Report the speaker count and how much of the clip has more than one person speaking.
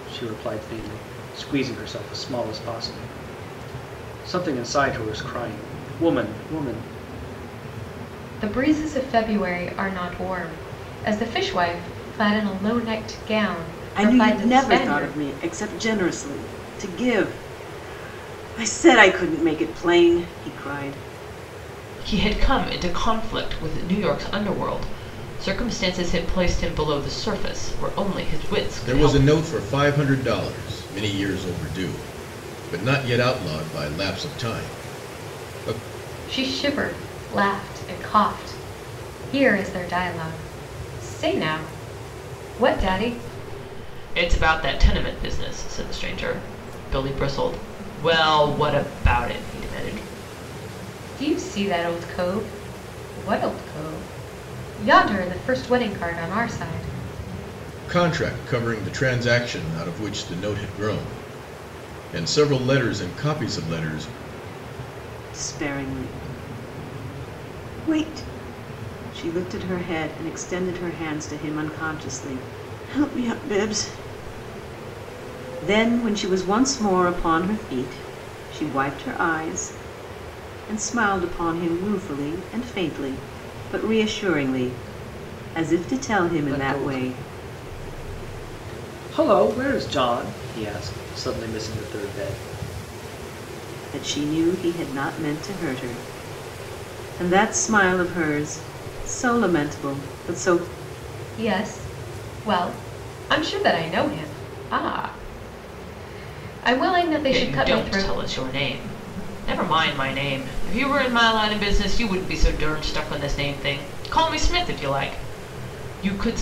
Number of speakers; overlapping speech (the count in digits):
5, about 3%